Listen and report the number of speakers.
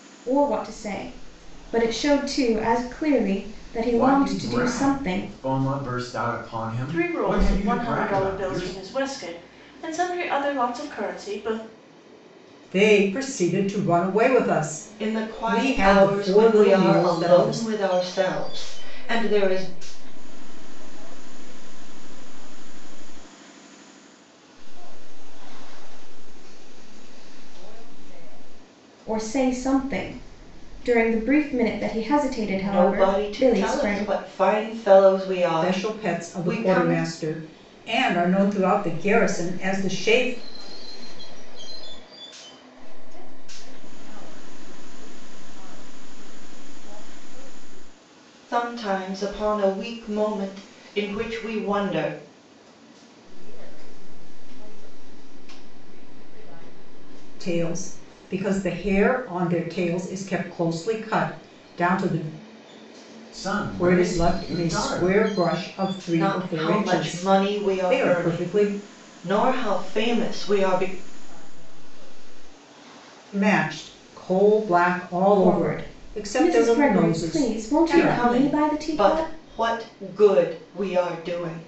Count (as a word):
six